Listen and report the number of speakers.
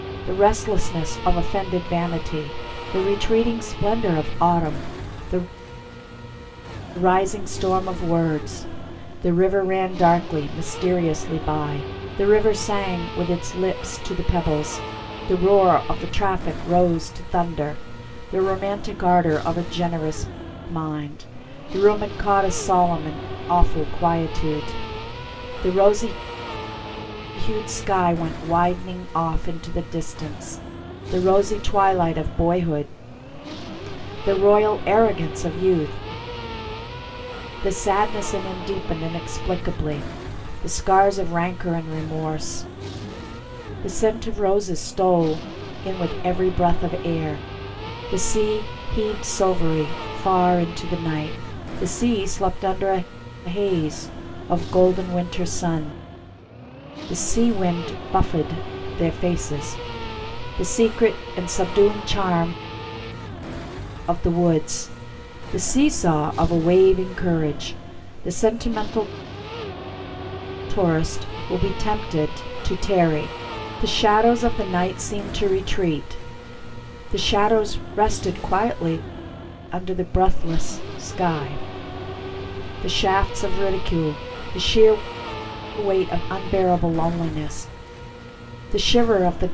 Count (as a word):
one